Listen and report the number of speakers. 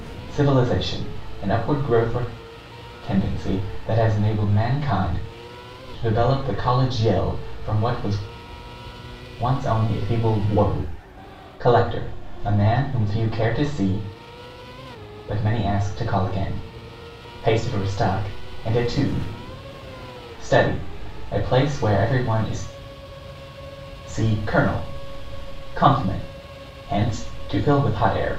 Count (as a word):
one